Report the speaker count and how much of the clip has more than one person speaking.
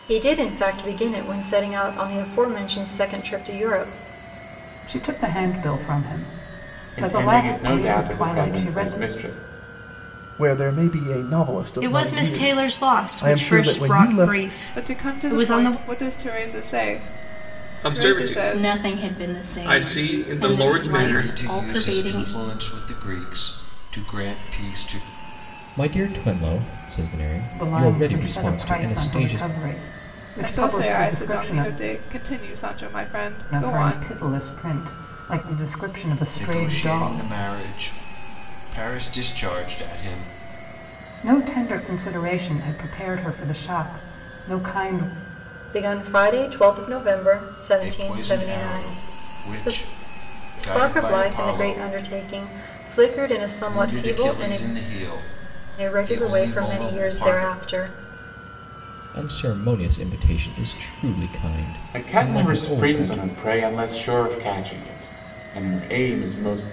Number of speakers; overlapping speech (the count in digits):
10, about 34%